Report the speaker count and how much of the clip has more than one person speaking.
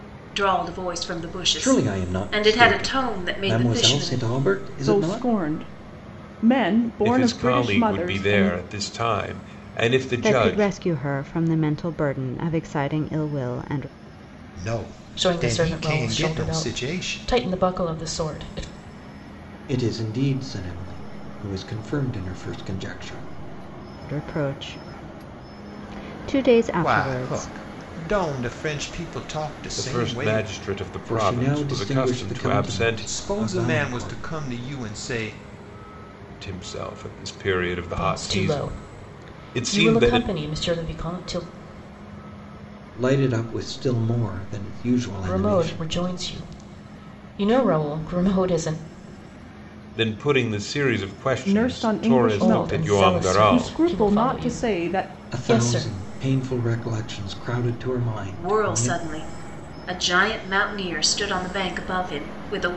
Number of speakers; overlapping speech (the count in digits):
7, about 32%